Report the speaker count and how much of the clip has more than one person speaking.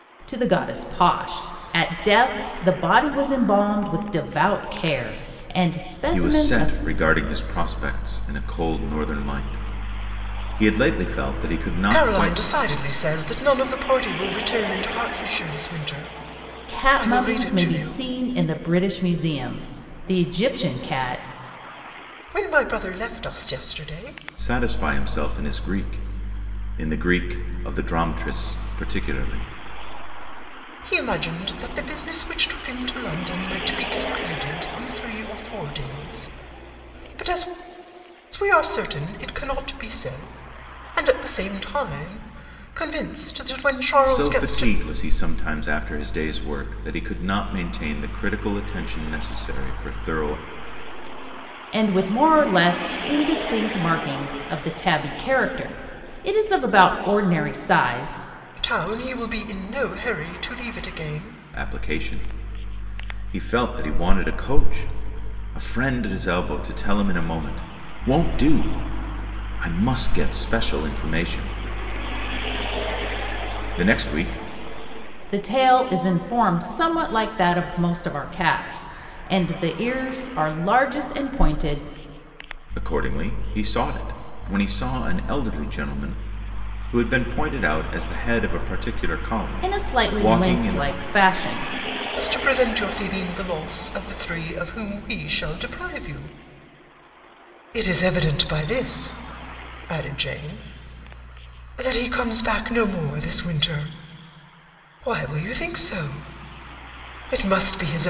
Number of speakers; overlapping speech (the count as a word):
three, about 4%